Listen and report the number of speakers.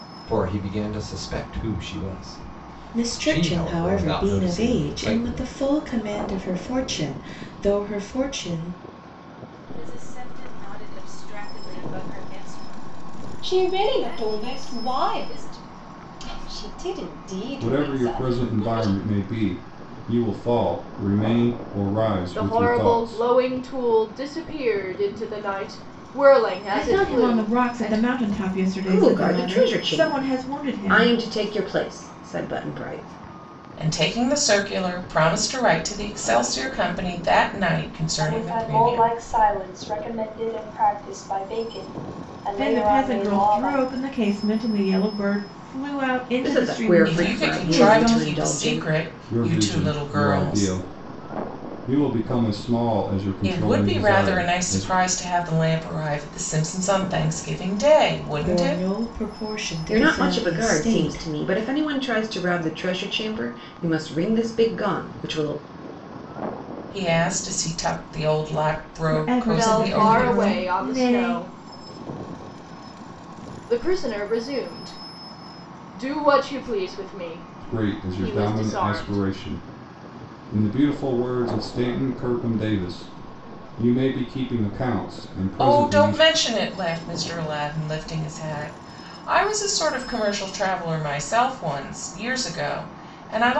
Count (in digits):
10